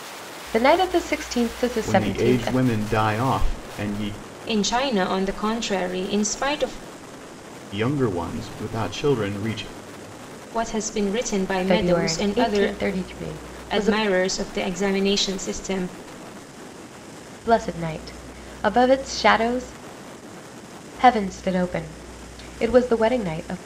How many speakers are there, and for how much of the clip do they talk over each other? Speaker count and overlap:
three, about 10%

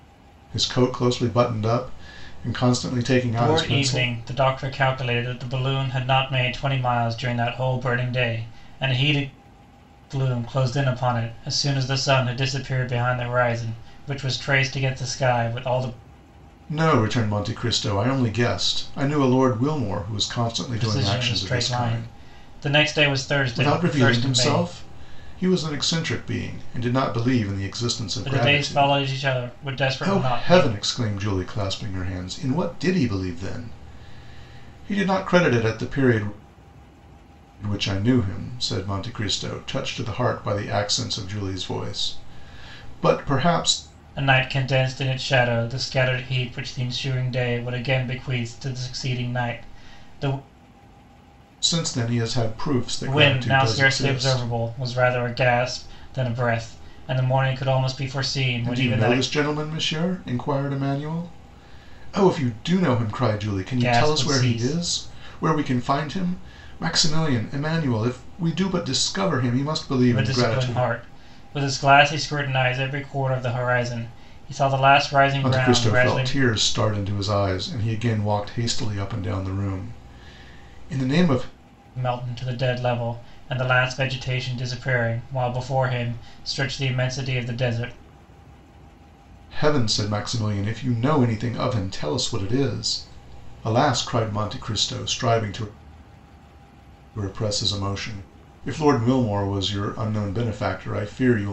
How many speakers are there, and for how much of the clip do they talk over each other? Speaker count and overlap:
two, about 10%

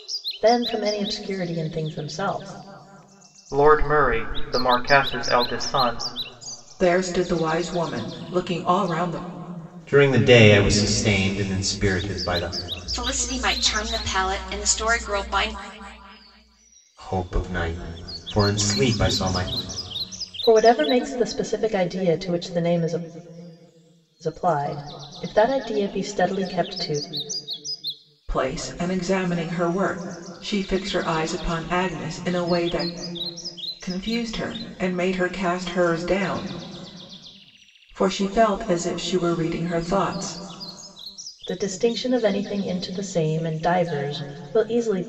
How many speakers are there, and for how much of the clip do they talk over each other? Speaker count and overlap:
five, no overlap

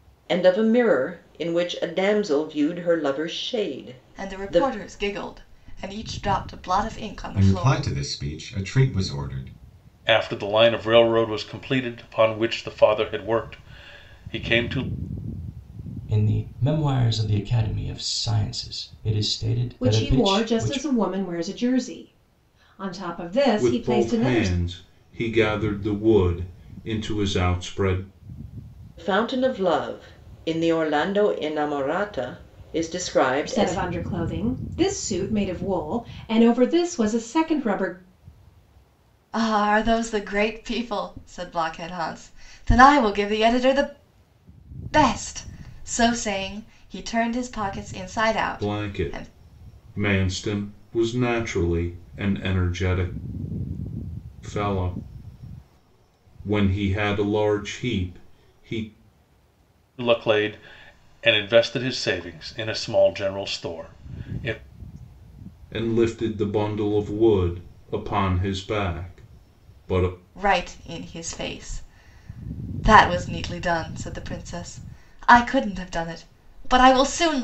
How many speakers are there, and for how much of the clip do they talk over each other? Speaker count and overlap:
seven, about 6%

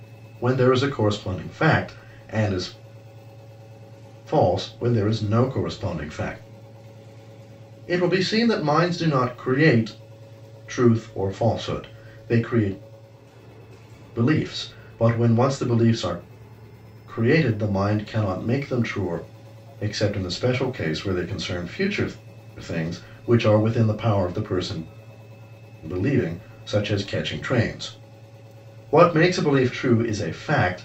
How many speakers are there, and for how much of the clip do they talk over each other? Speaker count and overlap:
one, no overlap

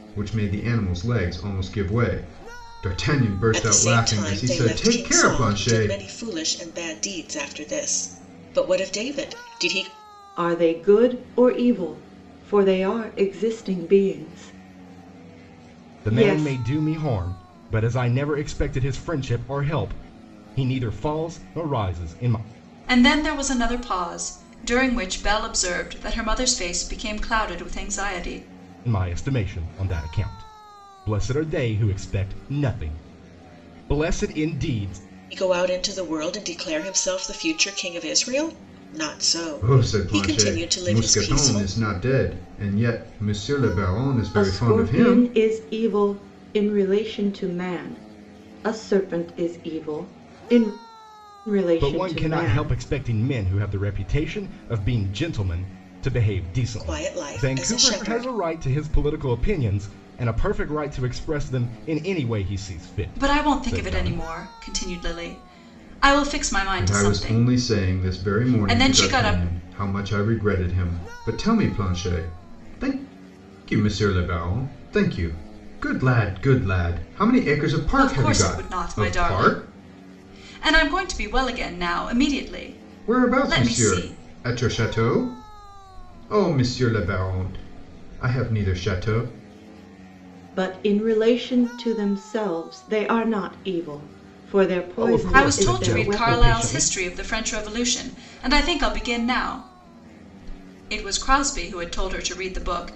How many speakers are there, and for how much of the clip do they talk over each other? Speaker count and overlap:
five, about 17%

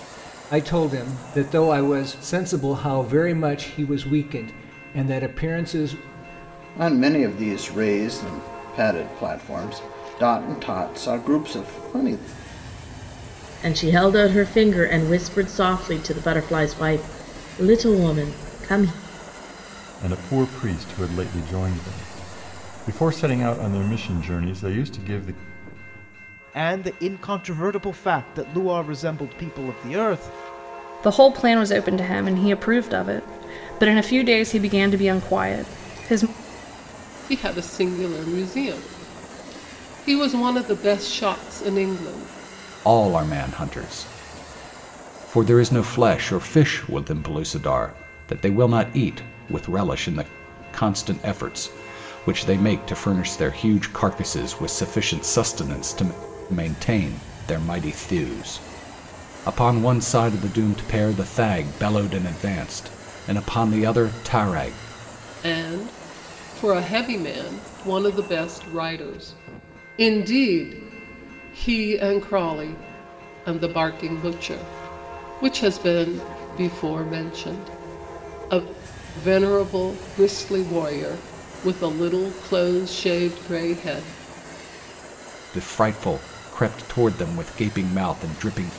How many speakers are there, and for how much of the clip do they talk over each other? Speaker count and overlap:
eight, no overlap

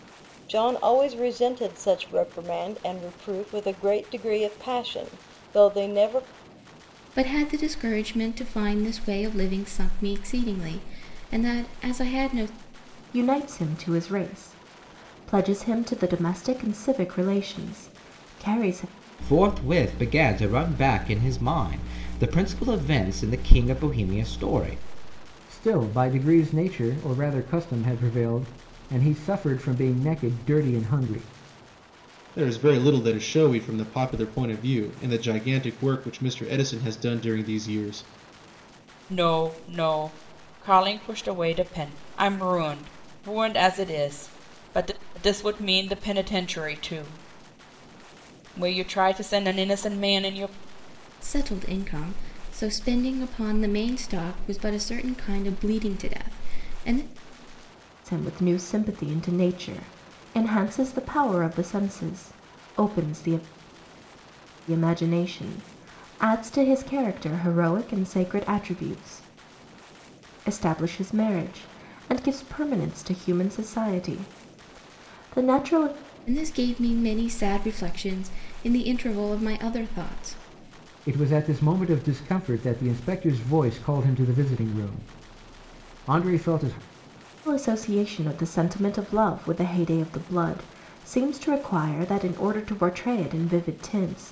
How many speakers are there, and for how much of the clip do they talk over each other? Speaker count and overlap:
seven, no overlap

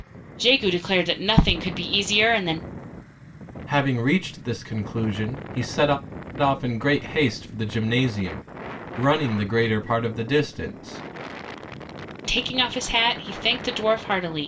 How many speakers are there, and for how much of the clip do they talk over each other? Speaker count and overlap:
two, no overlap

